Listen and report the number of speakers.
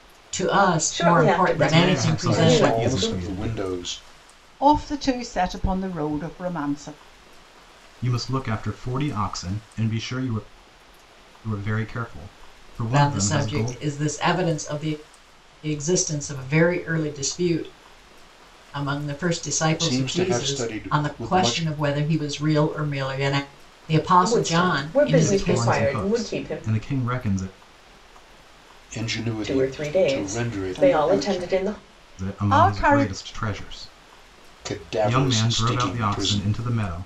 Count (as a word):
five